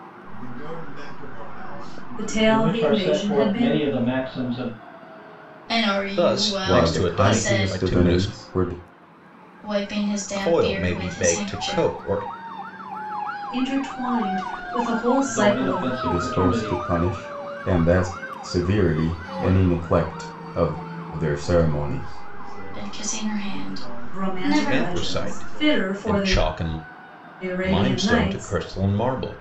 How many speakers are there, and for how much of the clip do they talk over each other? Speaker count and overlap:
6, about 42%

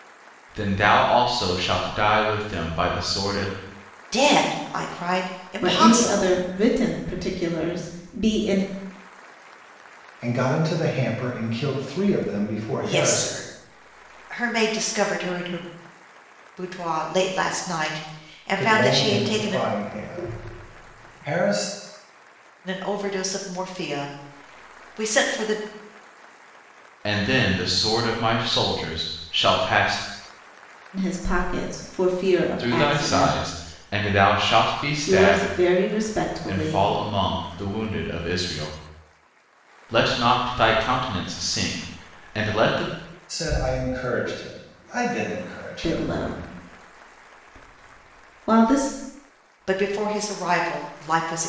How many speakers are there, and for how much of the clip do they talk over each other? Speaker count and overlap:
4, about 10%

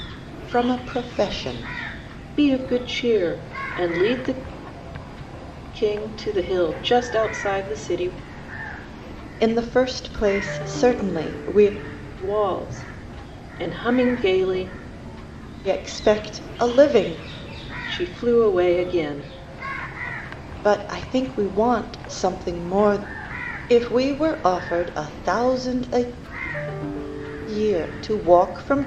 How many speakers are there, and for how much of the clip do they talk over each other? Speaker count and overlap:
2, no overlap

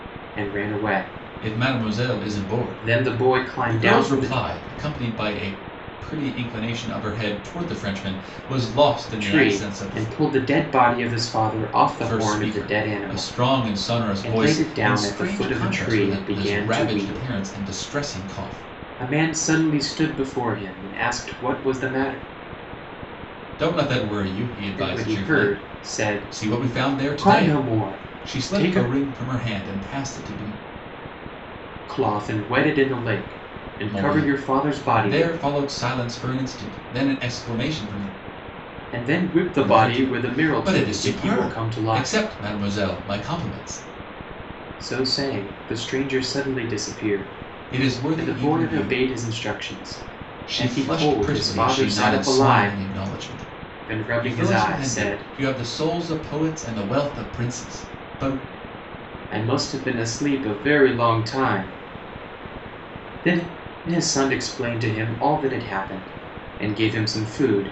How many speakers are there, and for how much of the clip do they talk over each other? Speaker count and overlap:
2, about 31%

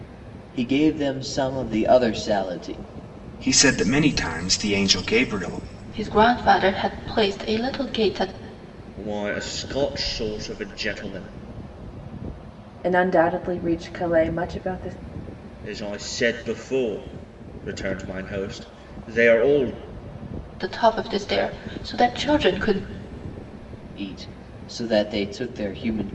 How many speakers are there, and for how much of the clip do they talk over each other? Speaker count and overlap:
5, no overlap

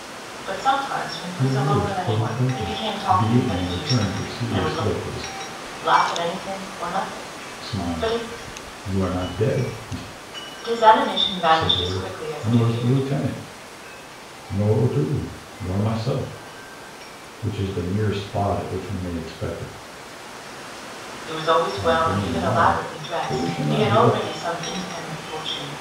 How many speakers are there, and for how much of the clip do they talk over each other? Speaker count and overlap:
2, about 30%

